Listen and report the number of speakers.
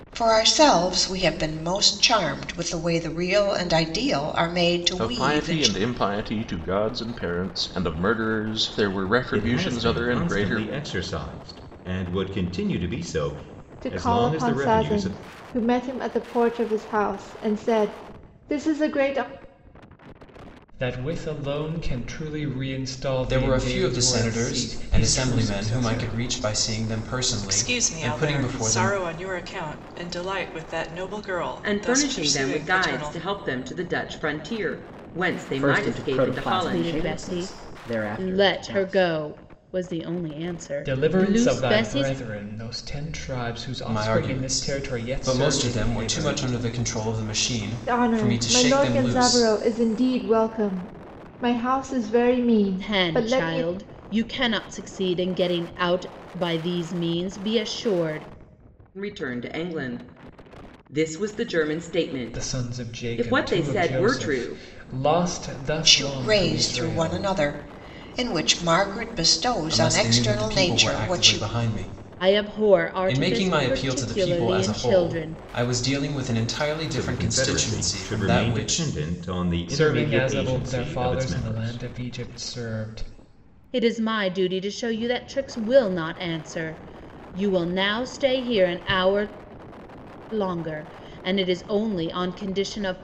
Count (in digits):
10